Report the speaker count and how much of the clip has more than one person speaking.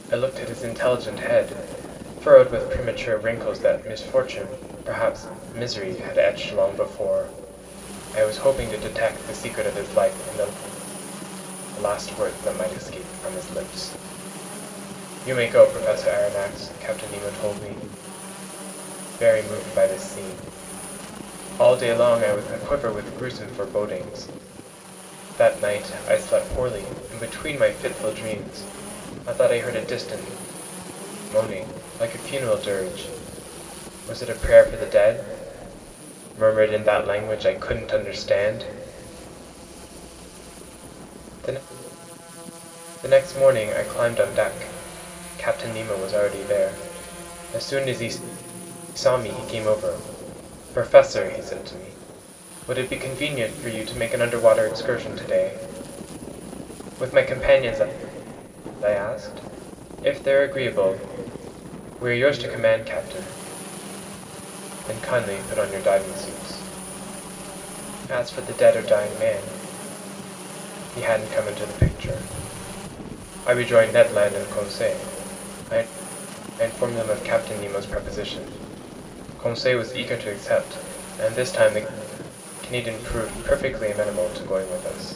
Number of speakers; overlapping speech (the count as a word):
one, no overlap